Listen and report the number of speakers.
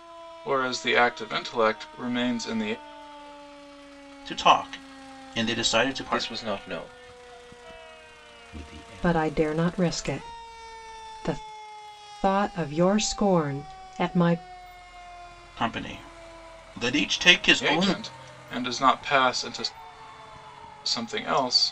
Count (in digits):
5